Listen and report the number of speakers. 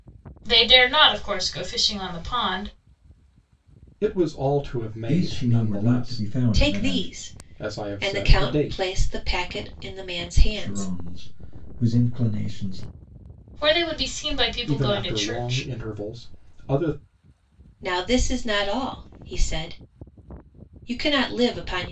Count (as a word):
four